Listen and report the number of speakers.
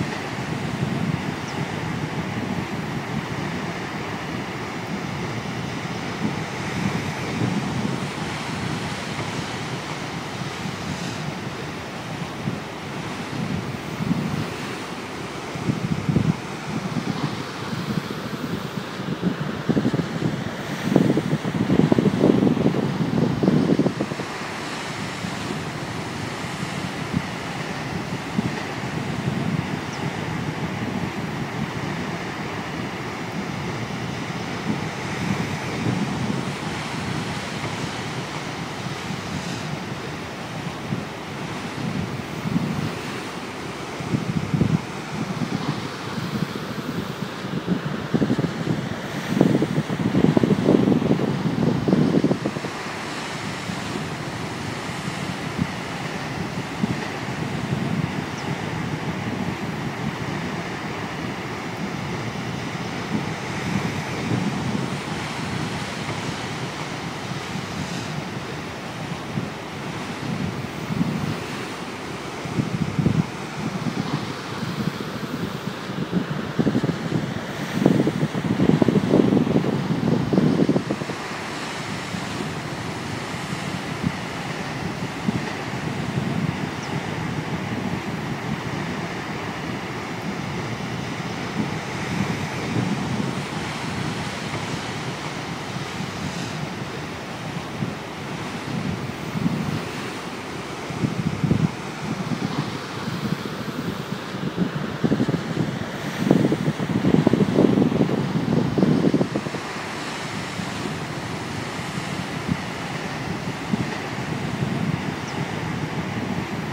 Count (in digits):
0